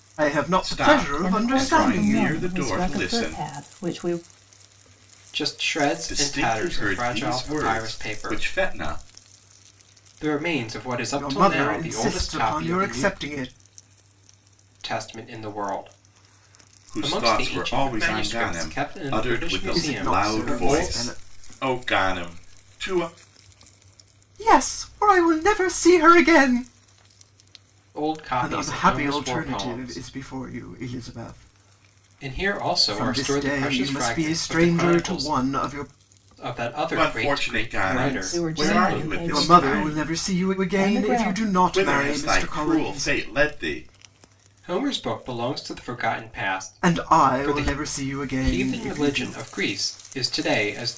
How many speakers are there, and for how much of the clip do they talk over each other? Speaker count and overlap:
four, about 46%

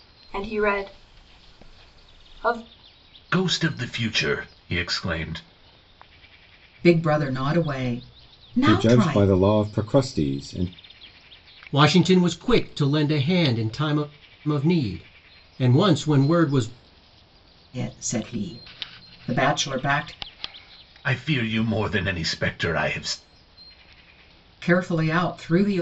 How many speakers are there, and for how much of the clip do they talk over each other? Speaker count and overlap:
five, about 3%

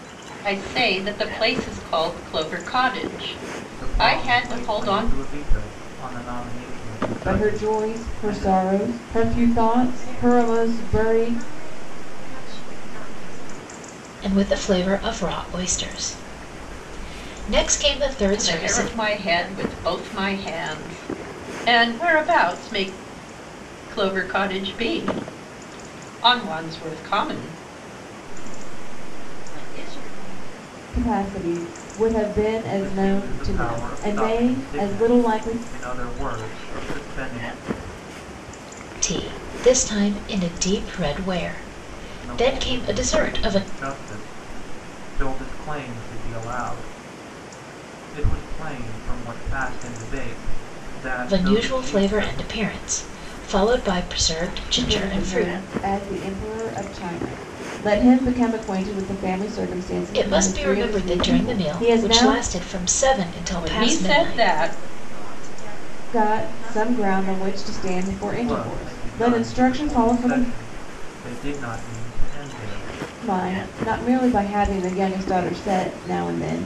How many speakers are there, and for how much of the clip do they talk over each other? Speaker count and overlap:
five, about 26%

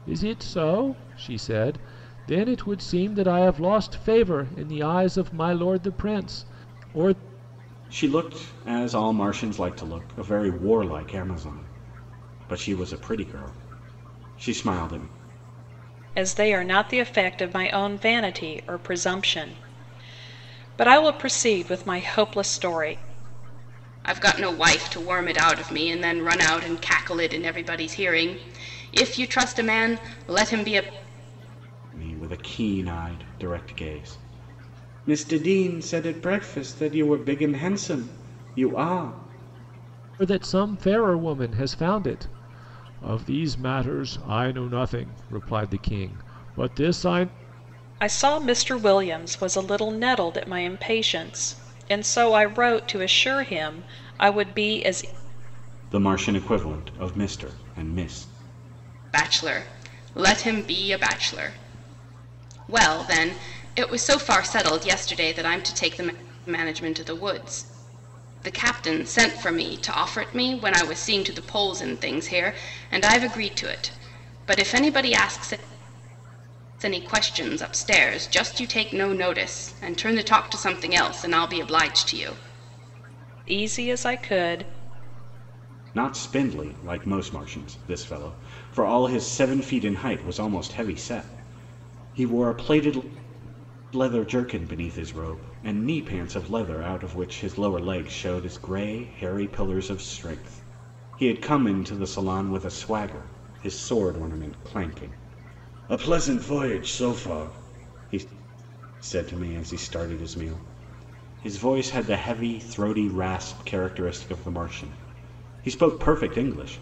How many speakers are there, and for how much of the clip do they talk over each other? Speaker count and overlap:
four, no overlap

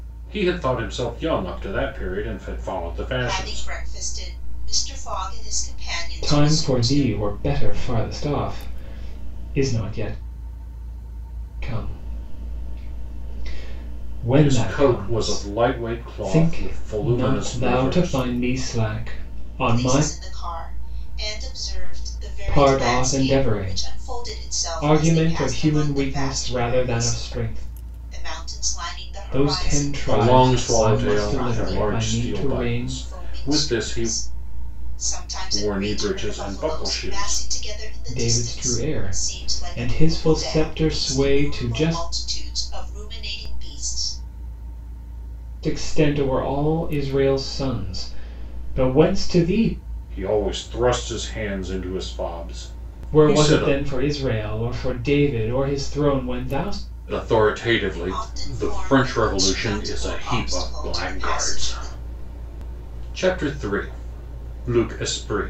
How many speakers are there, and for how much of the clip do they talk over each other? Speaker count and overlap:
three, about 37%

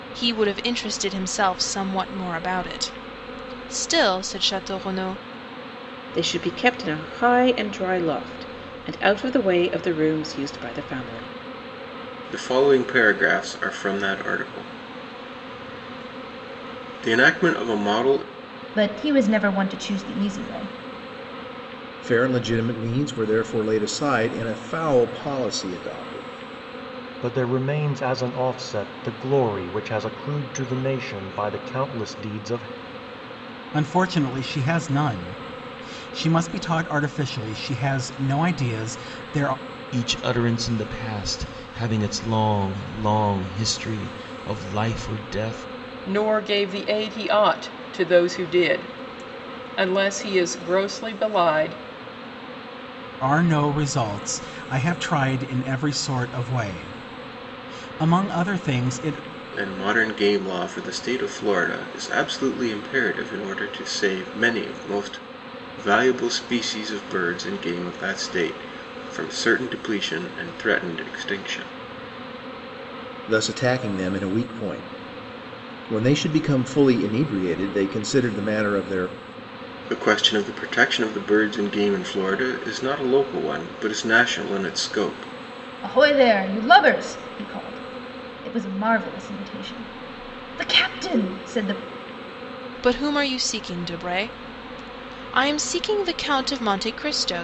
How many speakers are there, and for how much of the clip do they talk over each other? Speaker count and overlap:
nine, no overlap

